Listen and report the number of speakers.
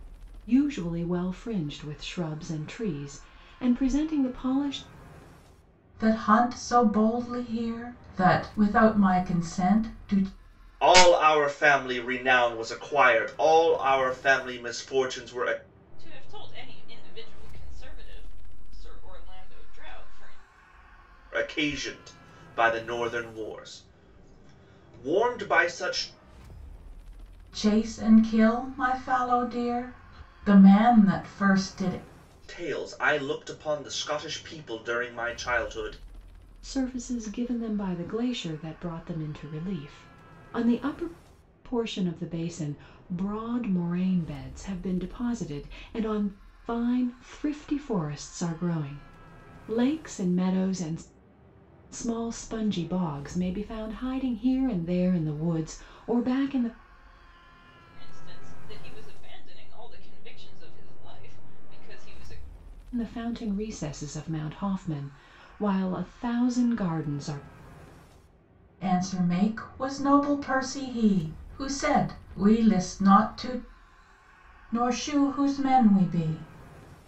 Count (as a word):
four